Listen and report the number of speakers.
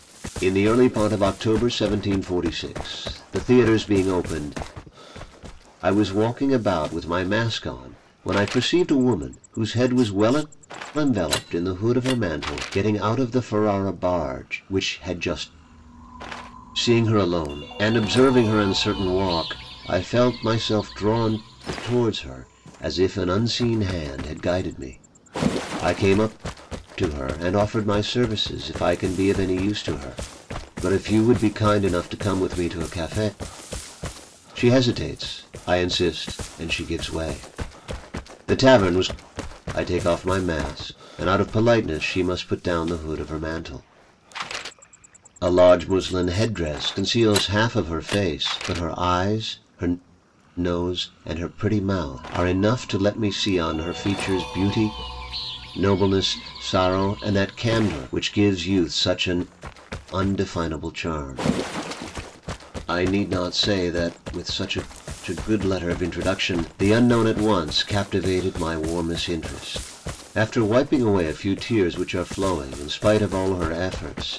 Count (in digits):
1